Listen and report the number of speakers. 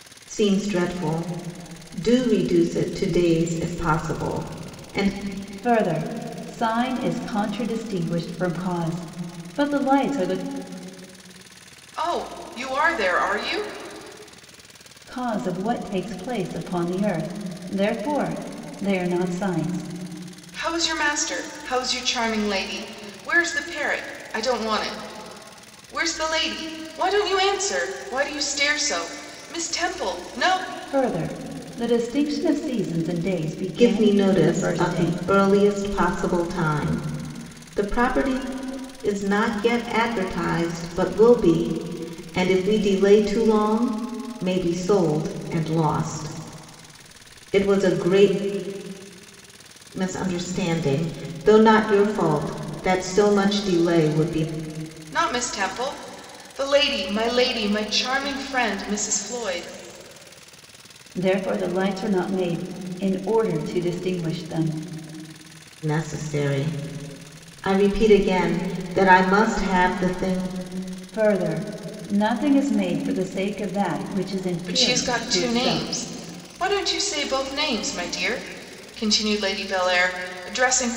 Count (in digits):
3